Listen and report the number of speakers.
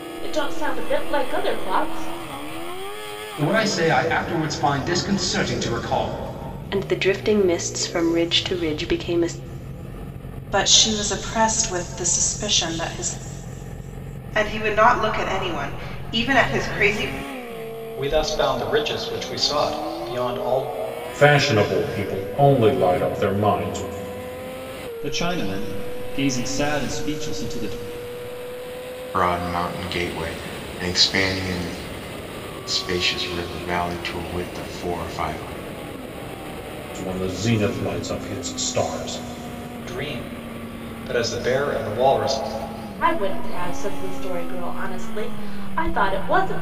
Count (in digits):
9